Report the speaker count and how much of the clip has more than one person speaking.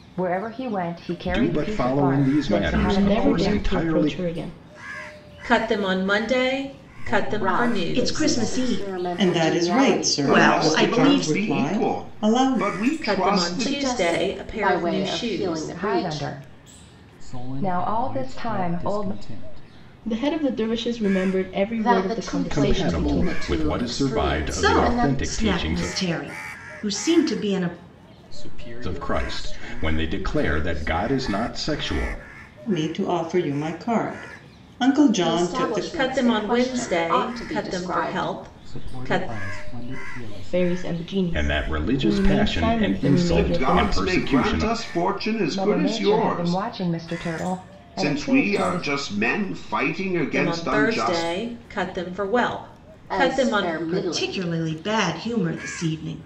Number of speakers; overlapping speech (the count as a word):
nine, about 57%